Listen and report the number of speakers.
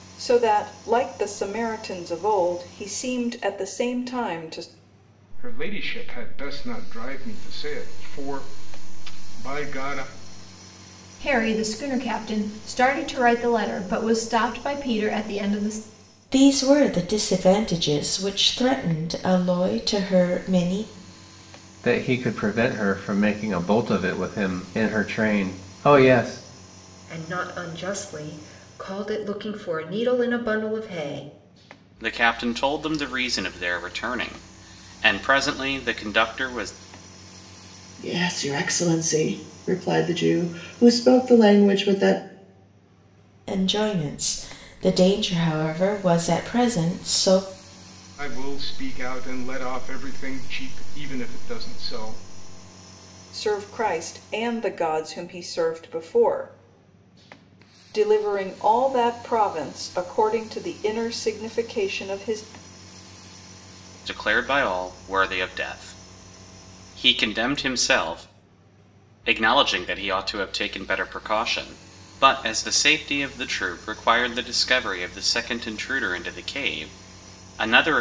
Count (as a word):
eight